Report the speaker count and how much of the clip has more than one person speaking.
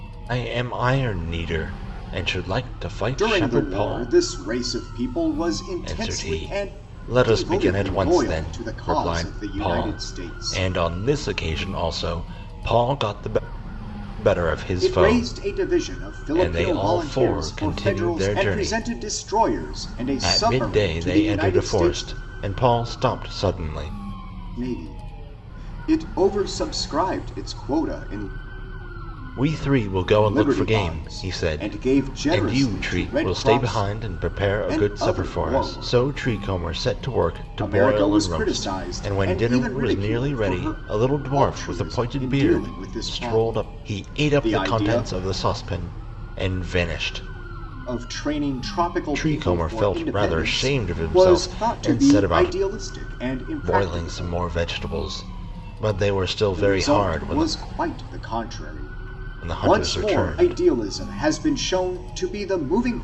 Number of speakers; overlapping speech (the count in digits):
2, about 45%